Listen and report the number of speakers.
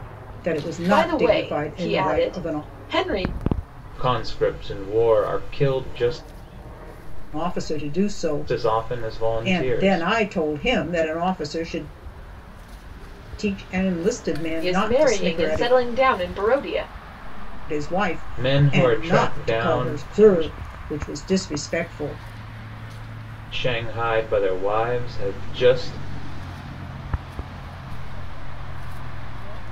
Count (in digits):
4